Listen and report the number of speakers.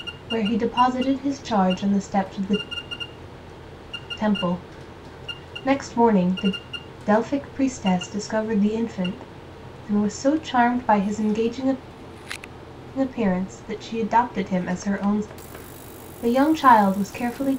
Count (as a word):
one